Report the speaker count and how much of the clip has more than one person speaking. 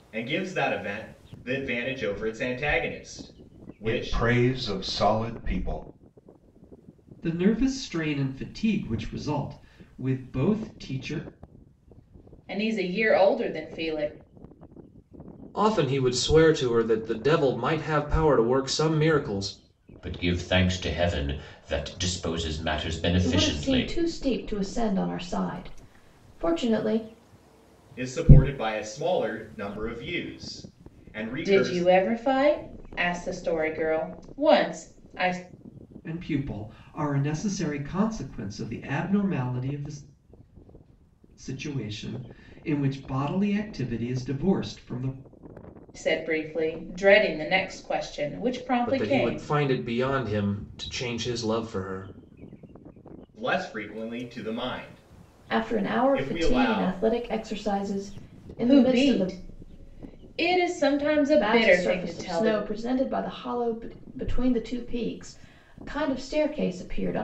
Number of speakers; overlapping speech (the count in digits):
7, about 9%